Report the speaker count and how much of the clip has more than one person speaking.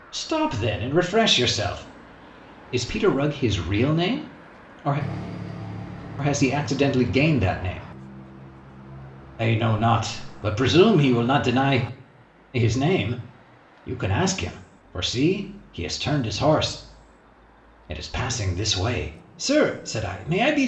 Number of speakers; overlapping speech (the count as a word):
one, no overlap